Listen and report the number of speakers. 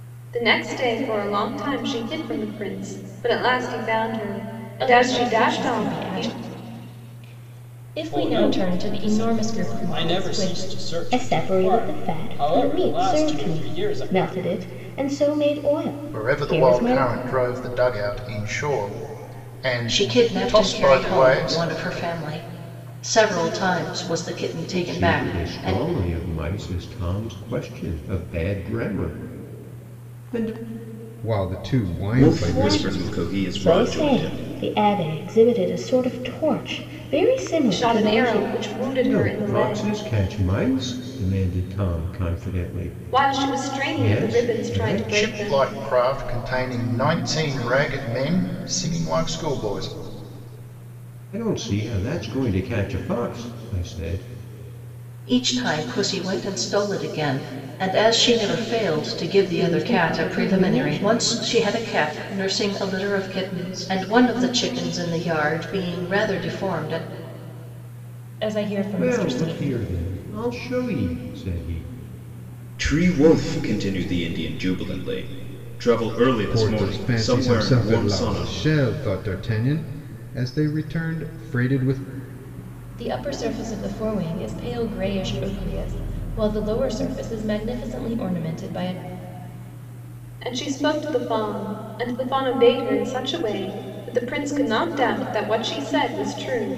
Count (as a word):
nine